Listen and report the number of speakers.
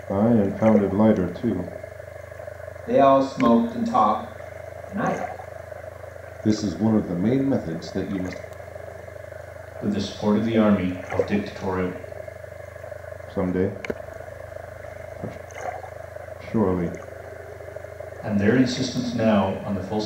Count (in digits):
4